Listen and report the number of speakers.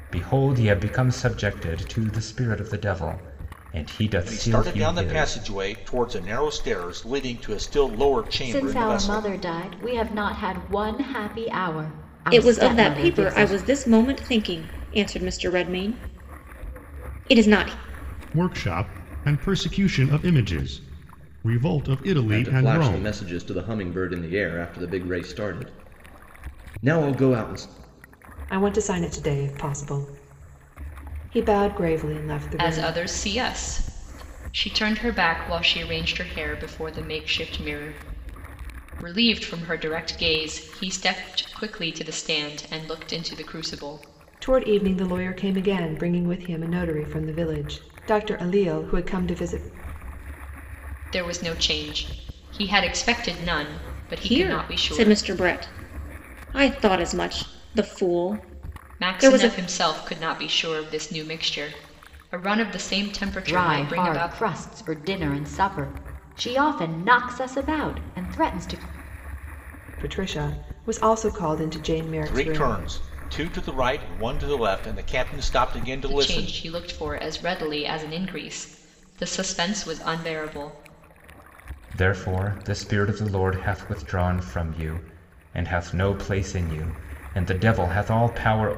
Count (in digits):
8